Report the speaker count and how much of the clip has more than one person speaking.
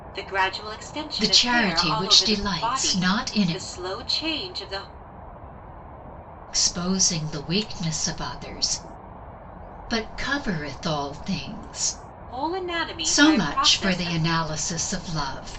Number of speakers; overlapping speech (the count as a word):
two, about 23%